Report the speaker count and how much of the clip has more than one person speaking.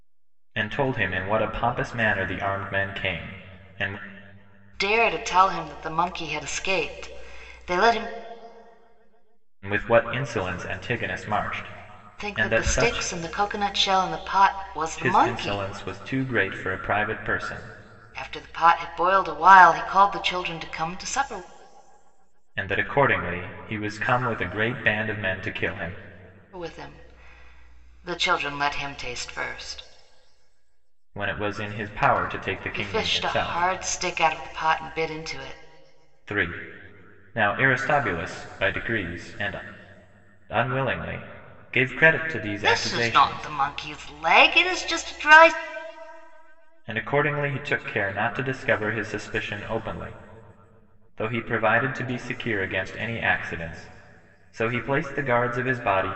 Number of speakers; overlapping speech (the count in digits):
2, about 6%